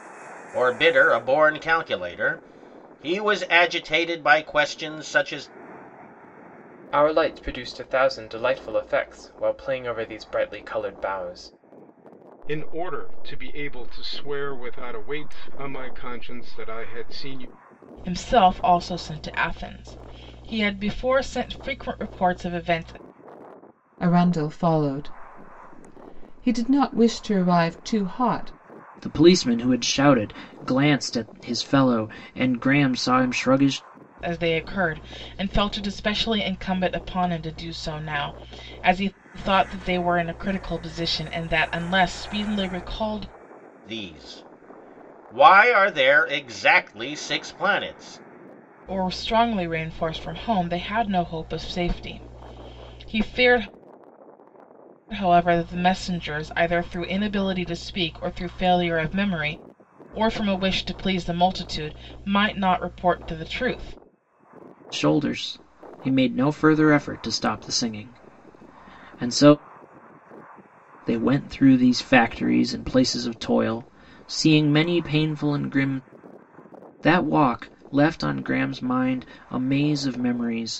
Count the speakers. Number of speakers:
6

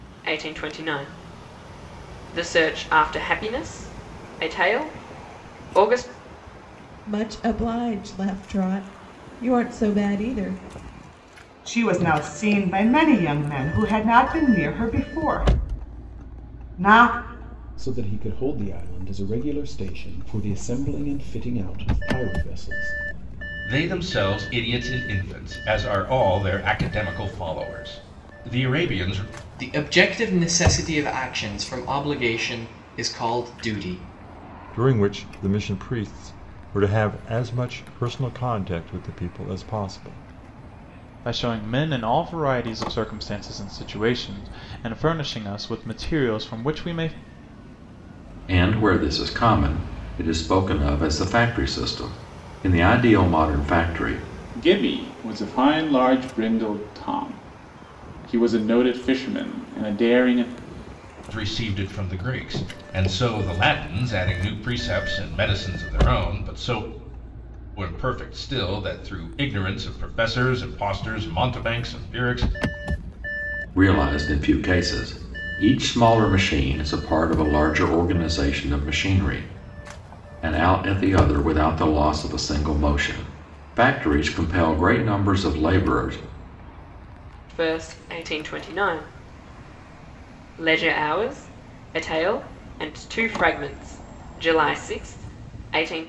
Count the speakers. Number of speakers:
10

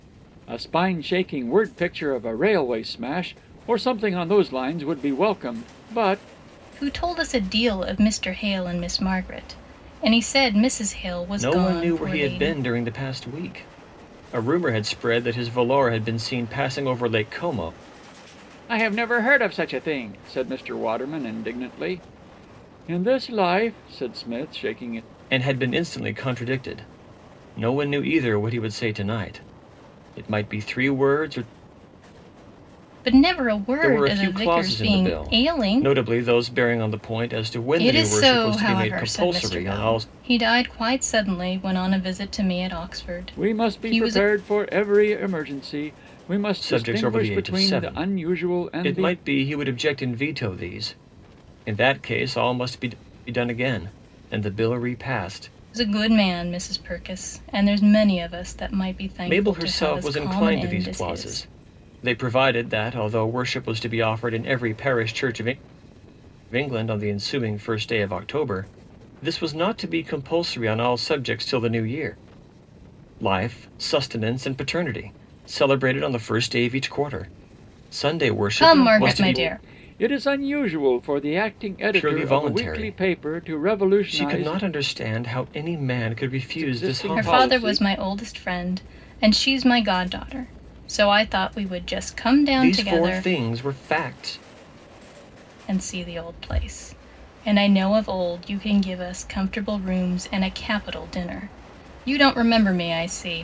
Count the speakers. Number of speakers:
3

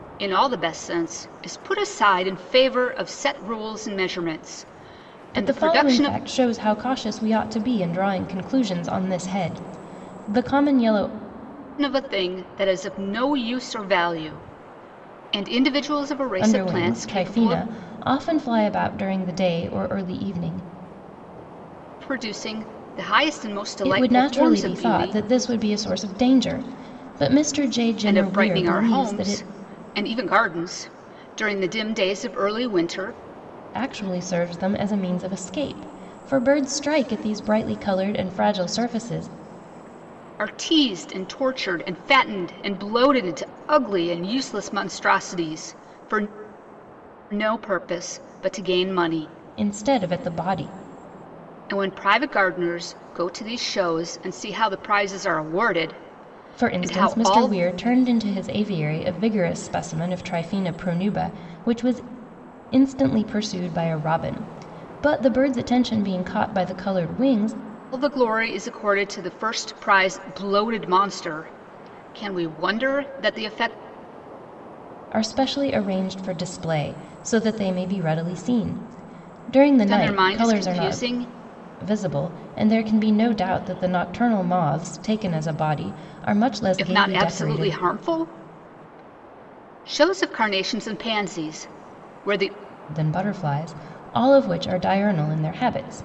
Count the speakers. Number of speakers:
2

